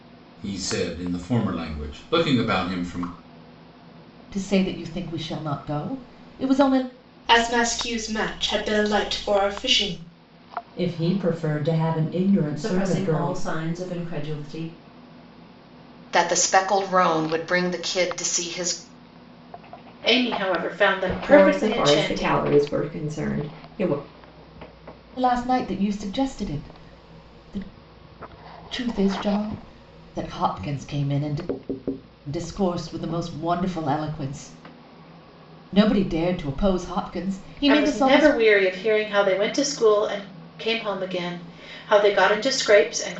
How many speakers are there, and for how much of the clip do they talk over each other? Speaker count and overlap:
8, about 6%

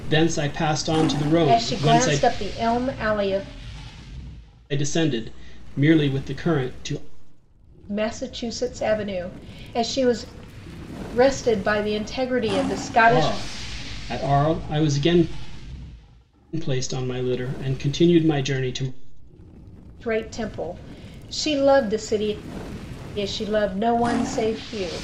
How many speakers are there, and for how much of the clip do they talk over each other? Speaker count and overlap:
2, about 4%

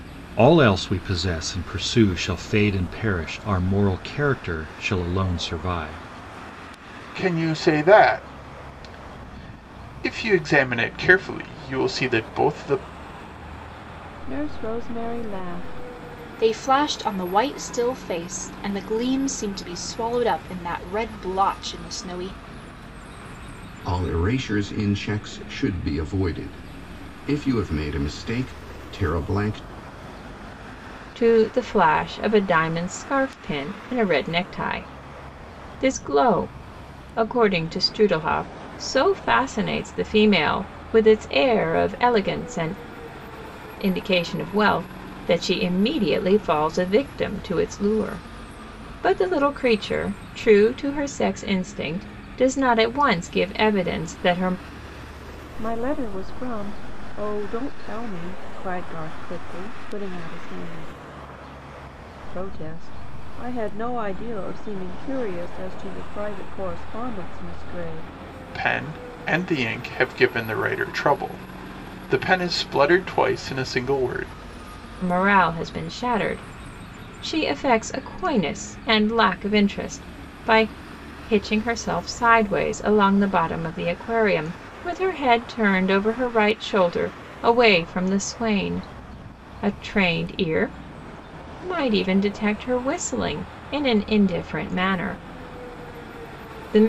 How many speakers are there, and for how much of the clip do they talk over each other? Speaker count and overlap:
6, no overlap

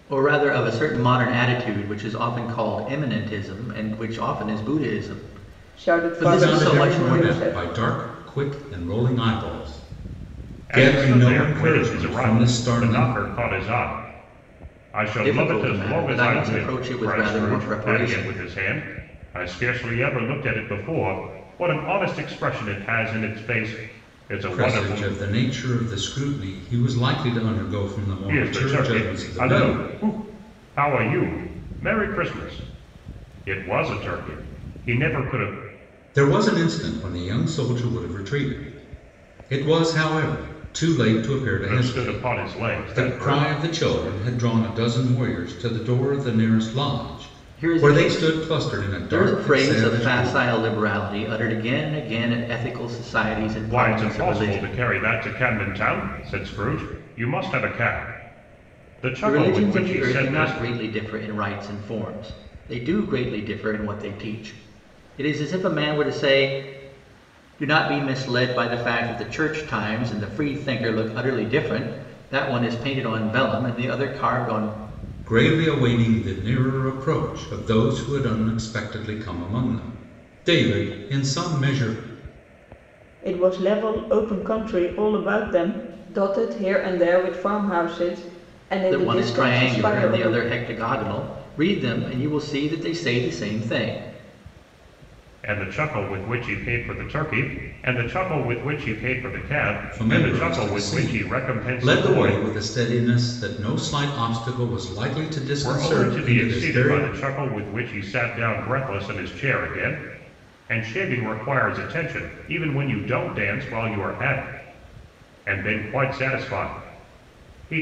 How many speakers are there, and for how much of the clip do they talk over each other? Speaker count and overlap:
4, about 19%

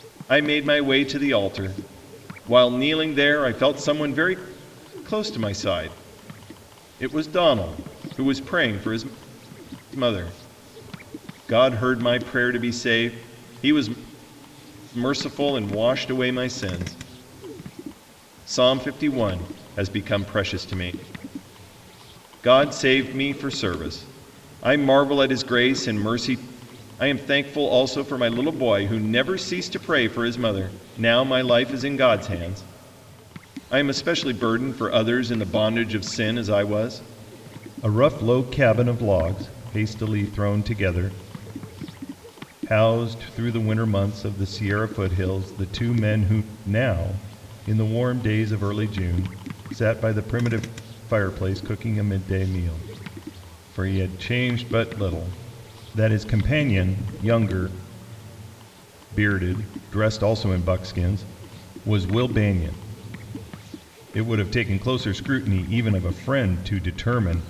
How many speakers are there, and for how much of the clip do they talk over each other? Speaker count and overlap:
1, no overlap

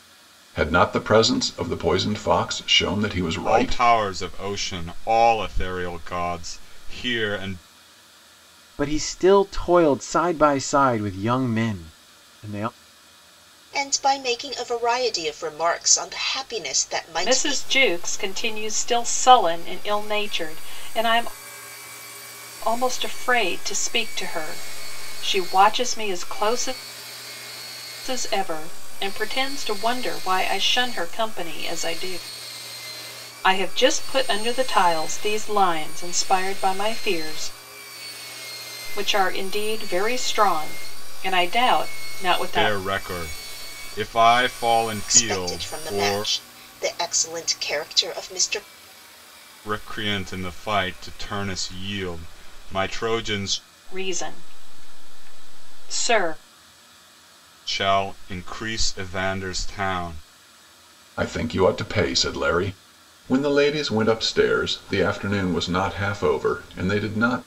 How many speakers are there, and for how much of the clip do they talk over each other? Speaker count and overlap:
5, about 4%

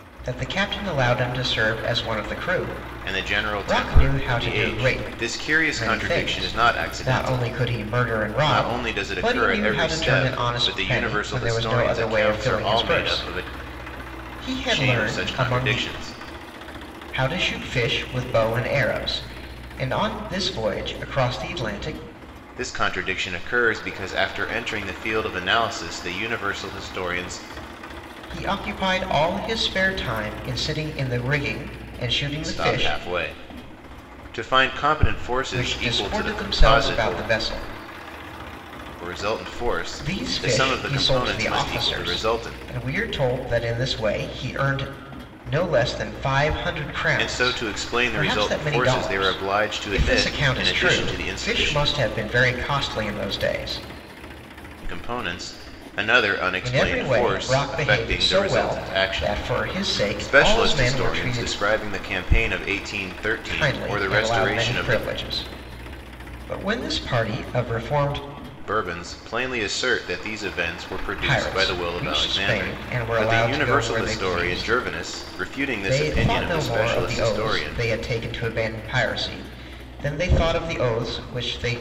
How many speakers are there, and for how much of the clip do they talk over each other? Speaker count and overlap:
2, about 38%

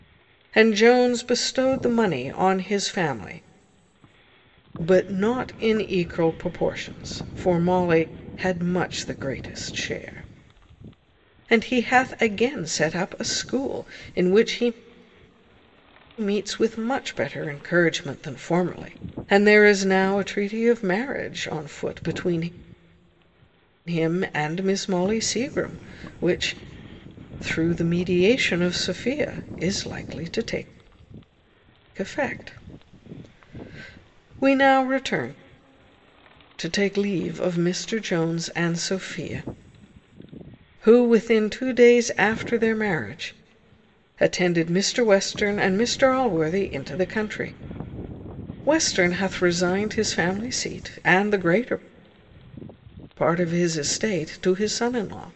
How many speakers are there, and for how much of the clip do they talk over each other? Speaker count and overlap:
1, no overlap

